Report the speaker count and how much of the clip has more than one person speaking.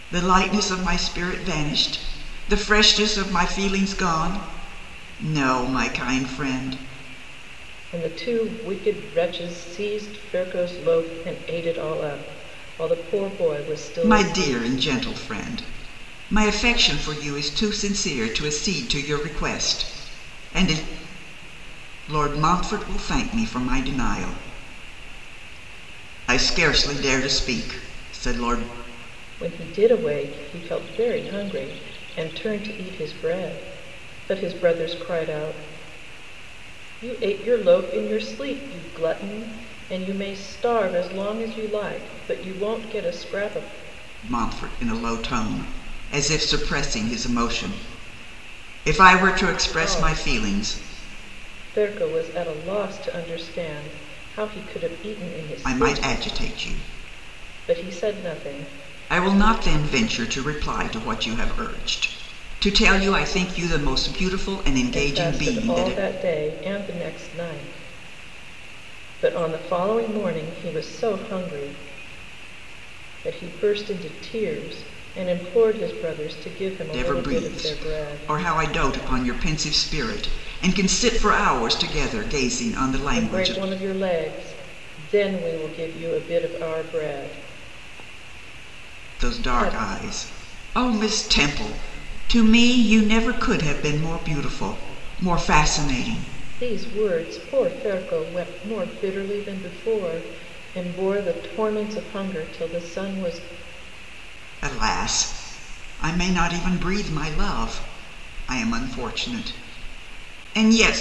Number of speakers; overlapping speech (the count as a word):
two, about 5%